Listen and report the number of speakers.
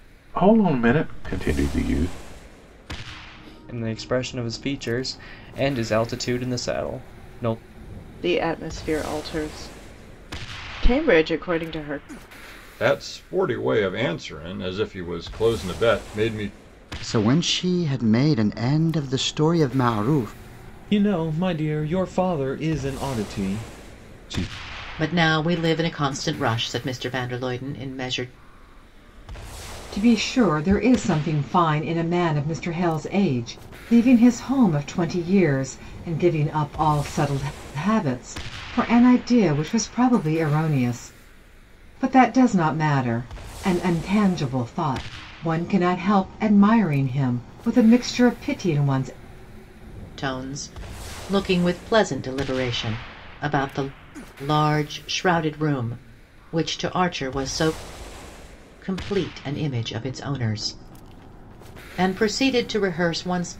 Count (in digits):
8